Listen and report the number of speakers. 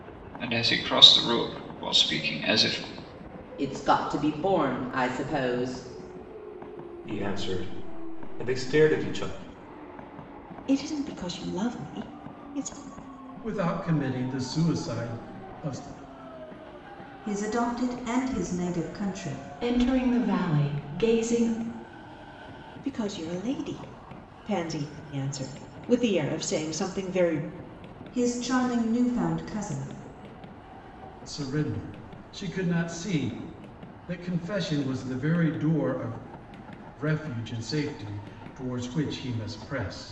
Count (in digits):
7